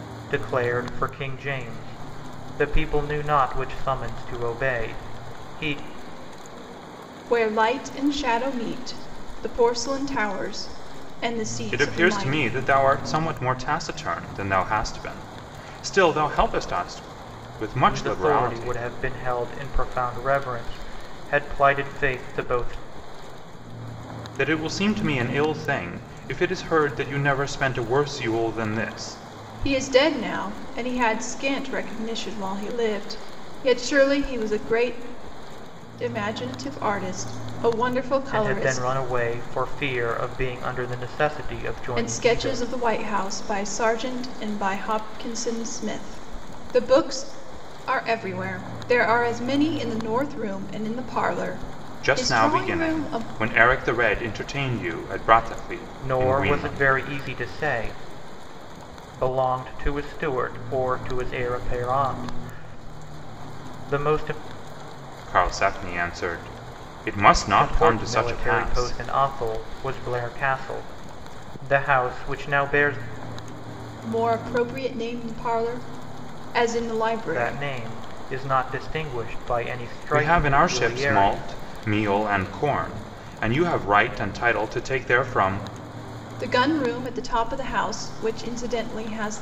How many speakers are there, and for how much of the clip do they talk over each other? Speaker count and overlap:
3, about 10%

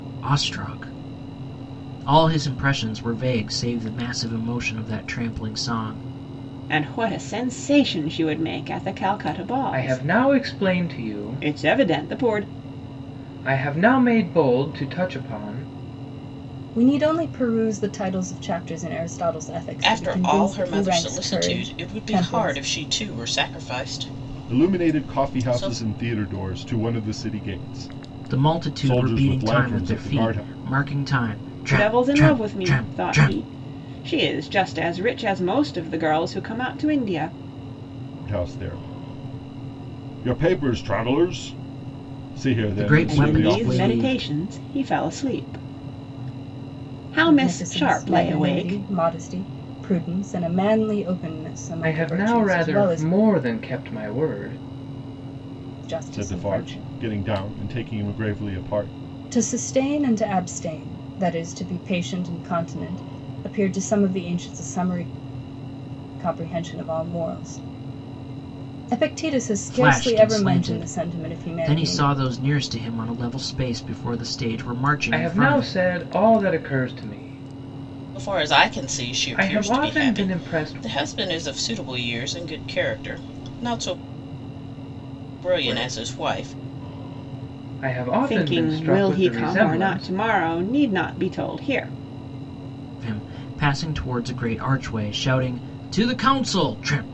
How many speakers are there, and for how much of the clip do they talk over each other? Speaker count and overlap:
6, about 26%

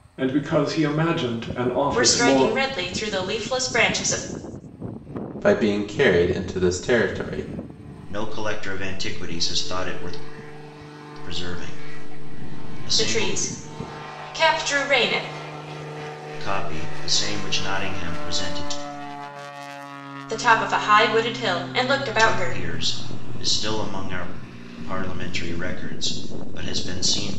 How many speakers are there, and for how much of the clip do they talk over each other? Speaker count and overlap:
4, about 6%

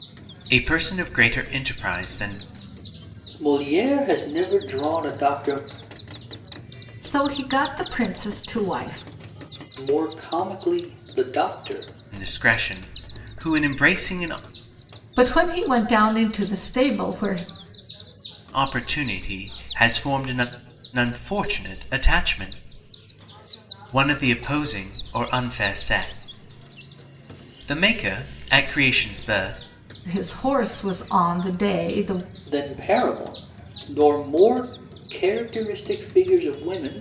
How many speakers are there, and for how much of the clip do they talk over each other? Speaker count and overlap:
3, no overlap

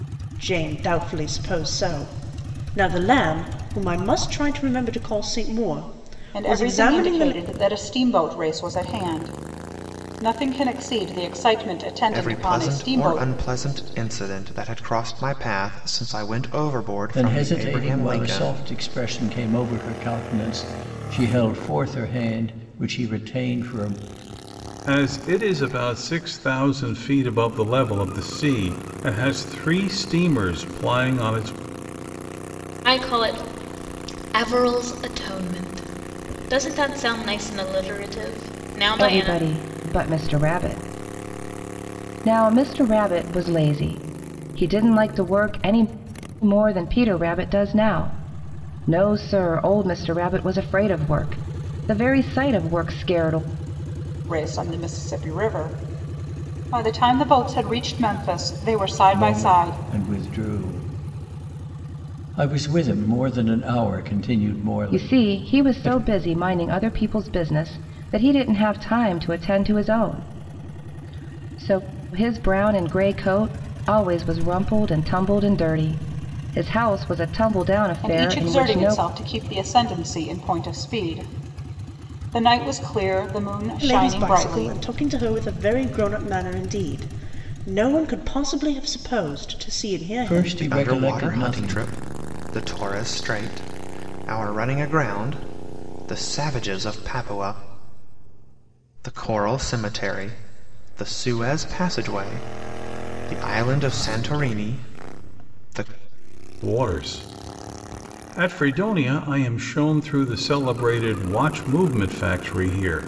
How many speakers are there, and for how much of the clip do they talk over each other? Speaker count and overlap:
7, about 9%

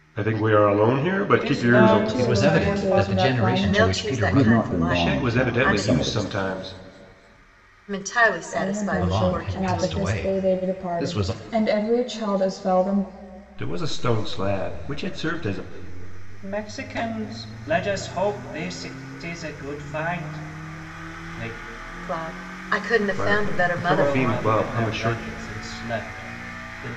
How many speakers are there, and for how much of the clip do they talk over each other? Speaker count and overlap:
6, about 37%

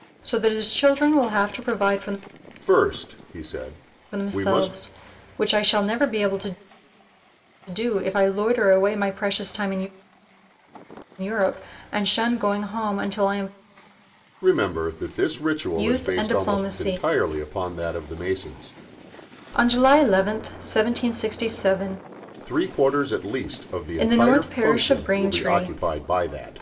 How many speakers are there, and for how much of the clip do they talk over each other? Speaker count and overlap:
2, about 14%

